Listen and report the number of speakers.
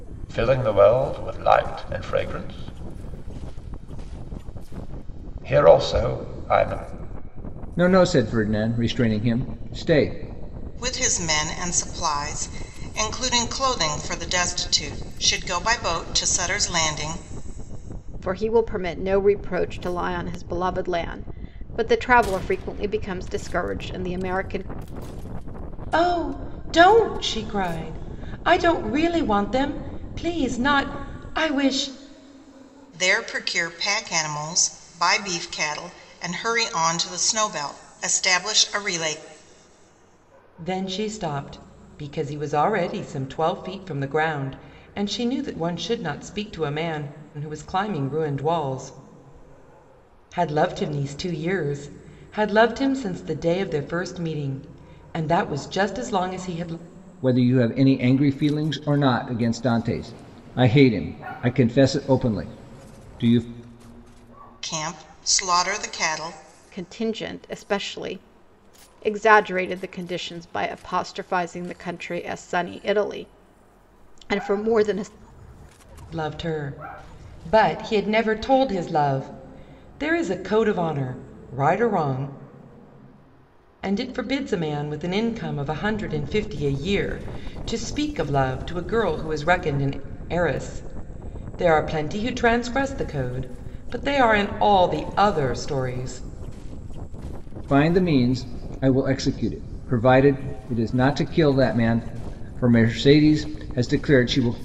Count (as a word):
five